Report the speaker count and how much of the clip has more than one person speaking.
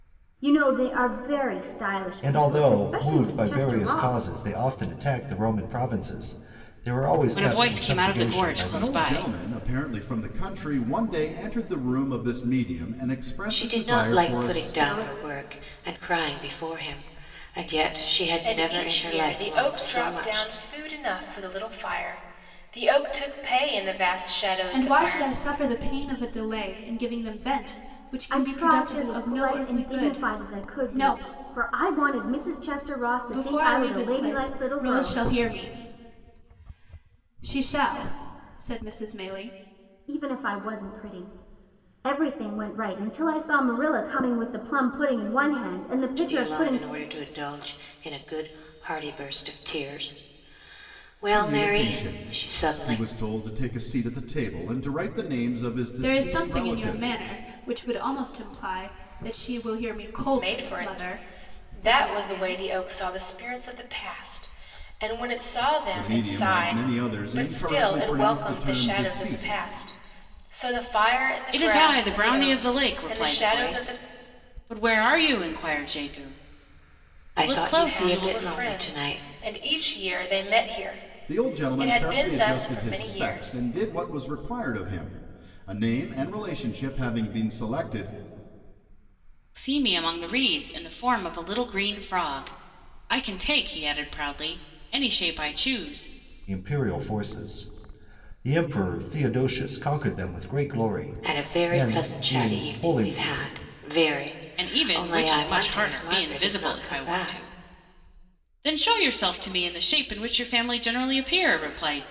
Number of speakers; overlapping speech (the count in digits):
7, about 31%